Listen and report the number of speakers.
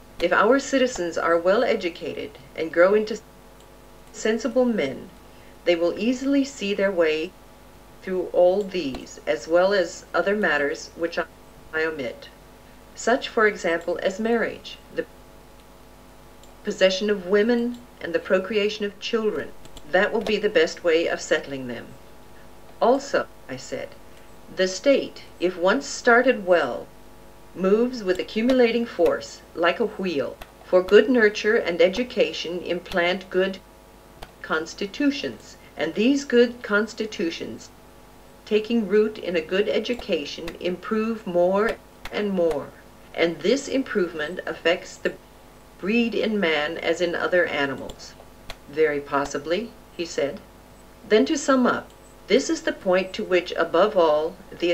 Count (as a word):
one